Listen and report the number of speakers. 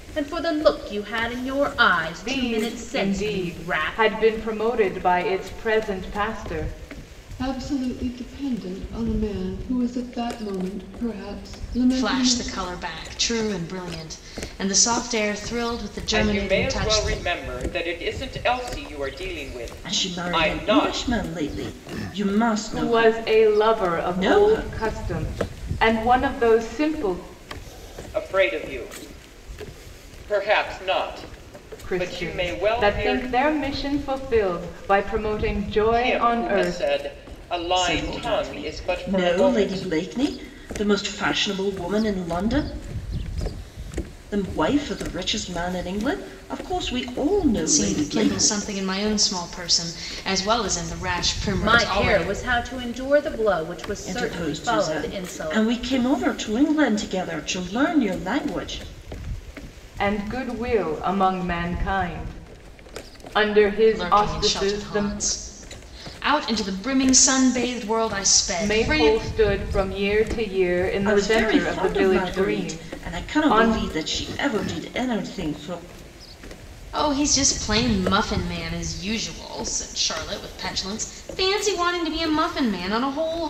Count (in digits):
6